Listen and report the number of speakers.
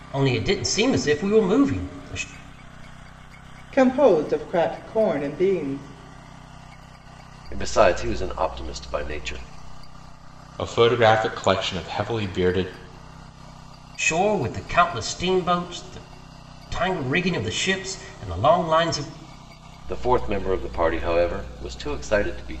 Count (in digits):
4